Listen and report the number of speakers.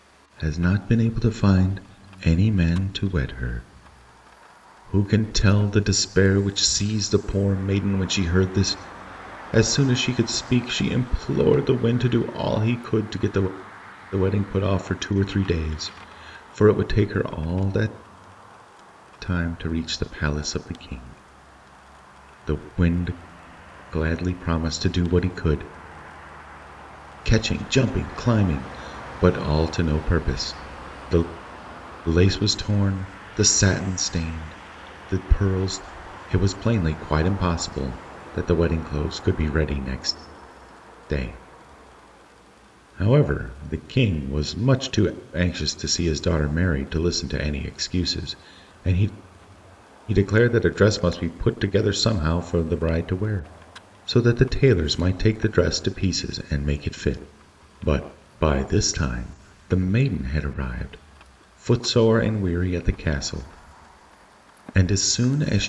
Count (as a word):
one